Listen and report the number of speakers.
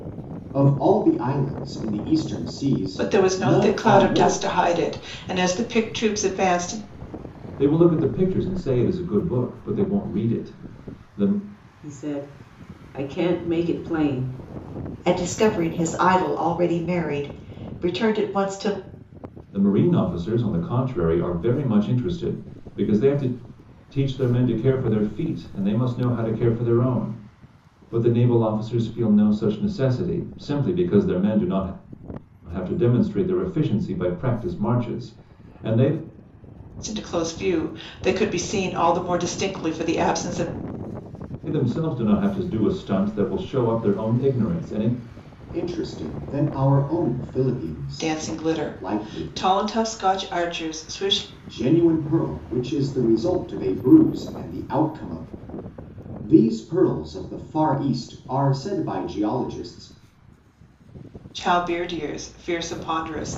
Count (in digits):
5